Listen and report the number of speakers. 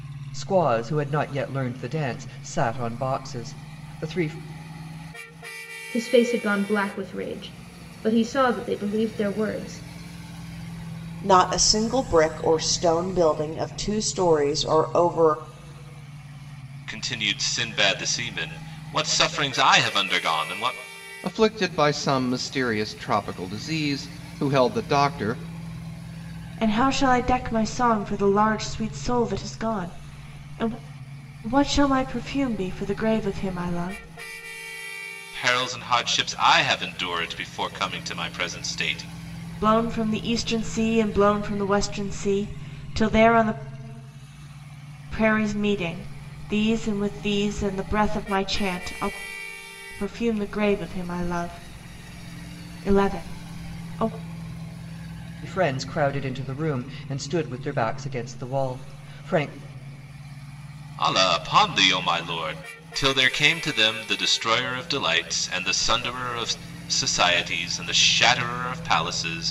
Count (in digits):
6